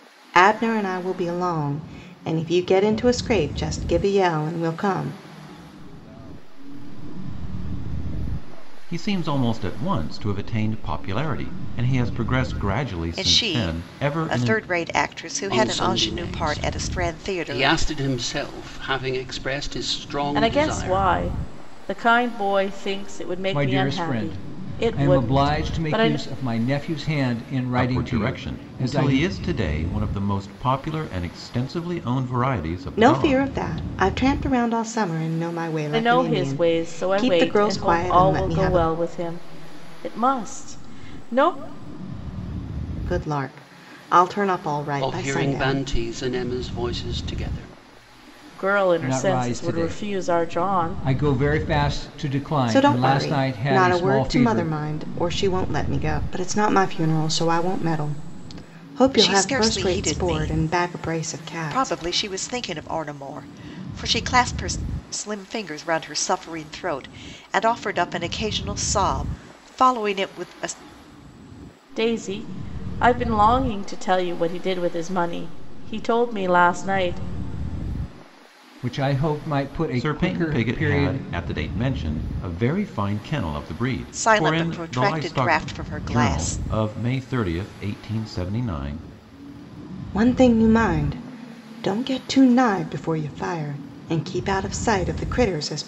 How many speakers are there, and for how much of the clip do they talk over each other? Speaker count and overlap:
7, about 31%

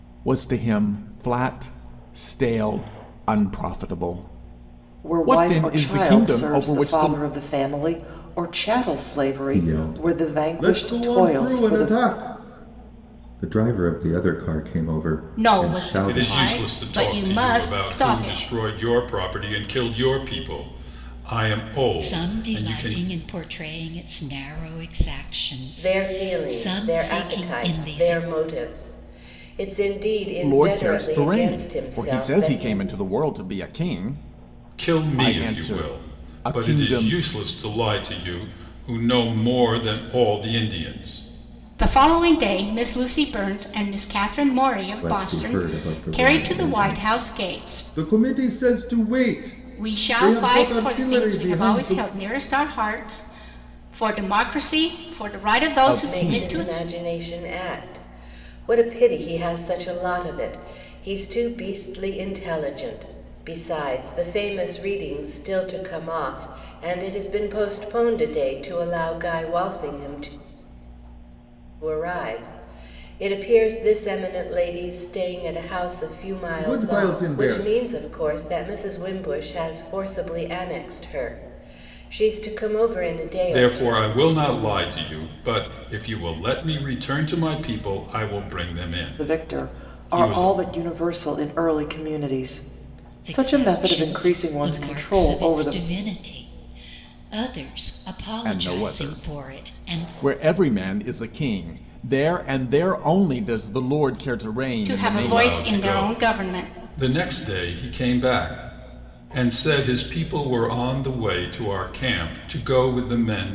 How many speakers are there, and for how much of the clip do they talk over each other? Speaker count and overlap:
7, about 28%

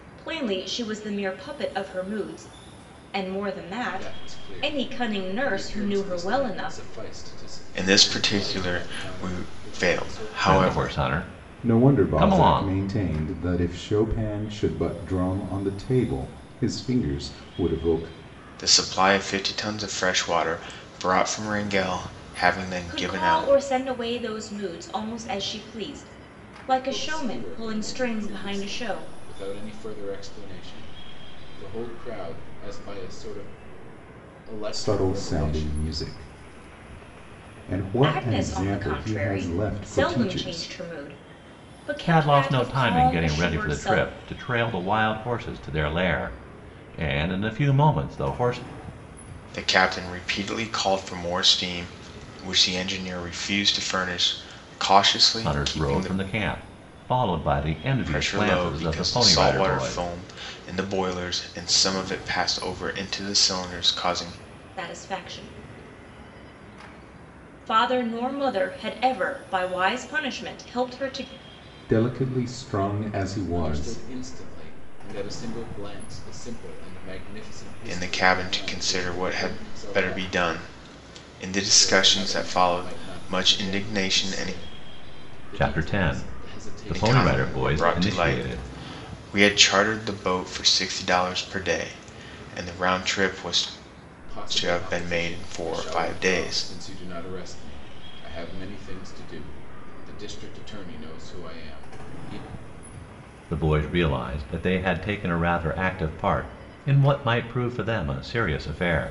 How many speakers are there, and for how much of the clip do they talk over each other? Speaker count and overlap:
5, about 28%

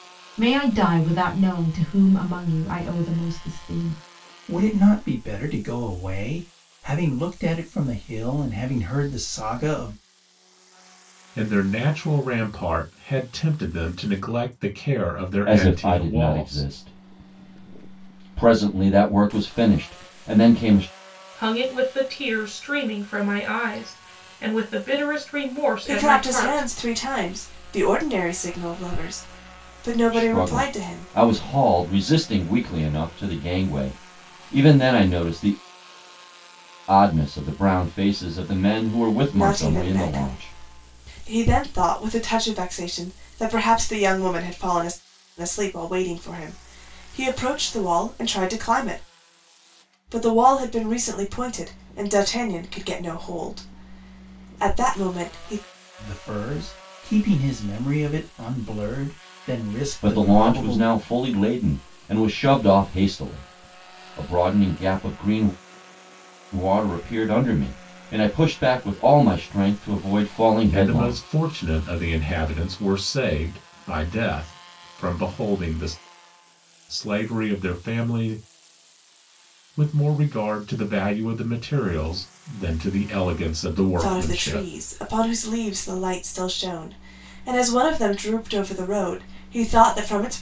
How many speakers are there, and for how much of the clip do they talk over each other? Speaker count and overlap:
6, about 7%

